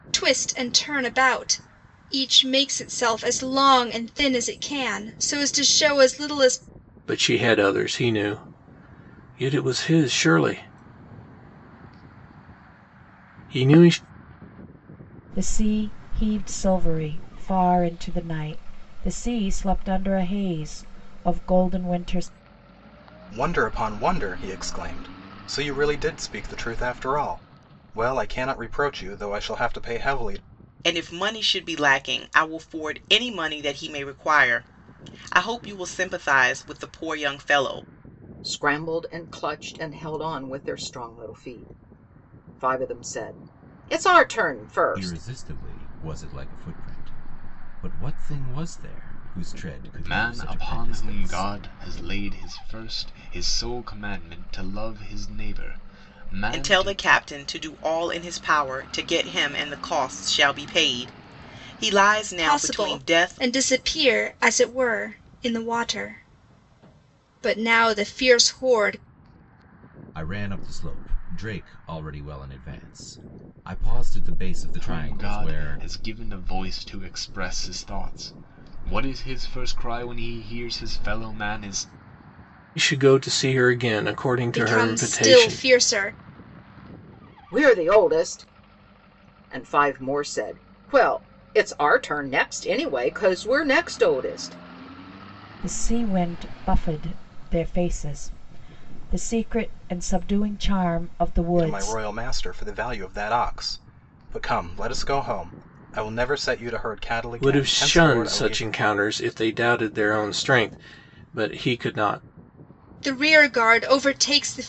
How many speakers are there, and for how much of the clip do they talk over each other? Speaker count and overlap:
eight, about 6%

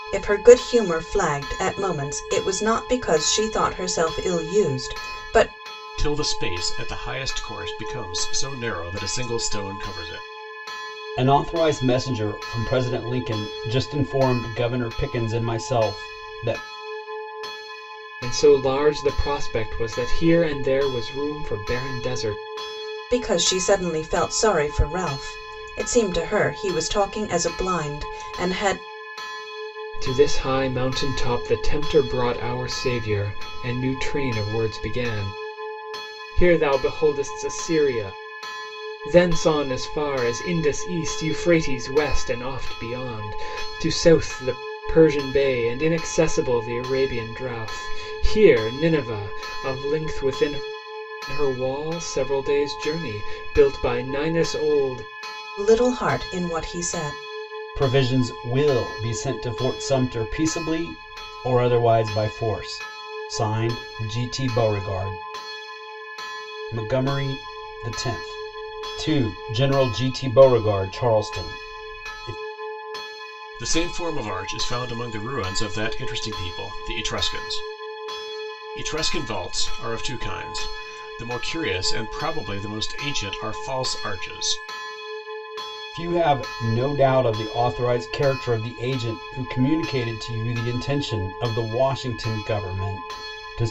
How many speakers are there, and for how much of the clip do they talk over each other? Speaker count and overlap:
four, no overlap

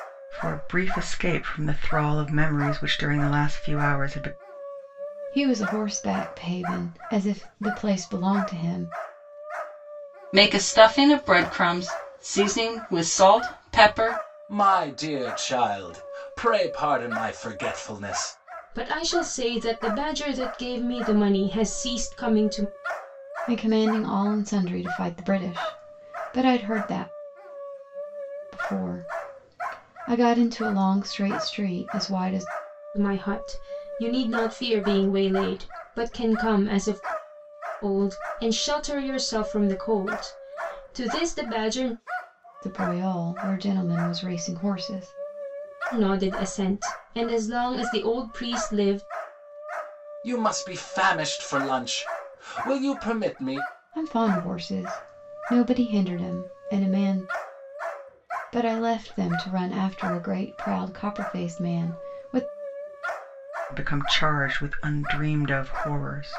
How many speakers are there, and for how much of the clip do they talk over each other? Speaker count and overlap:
five, no overlap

